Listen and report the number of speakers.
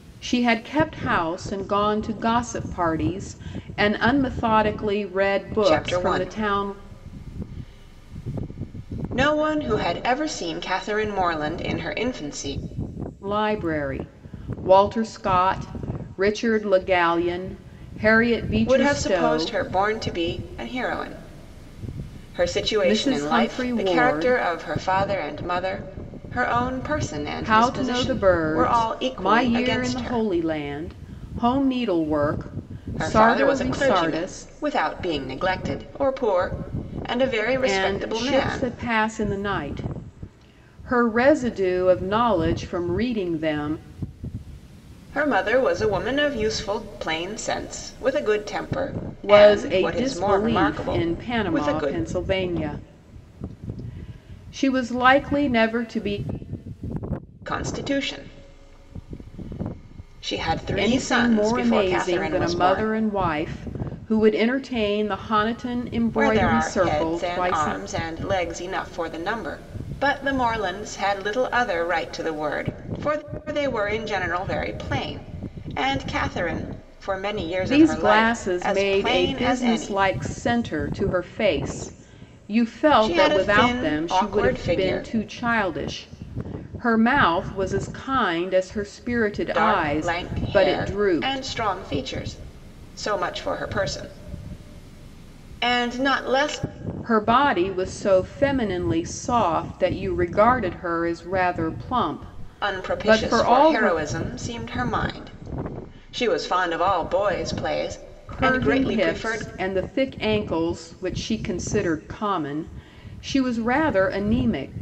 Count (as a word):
two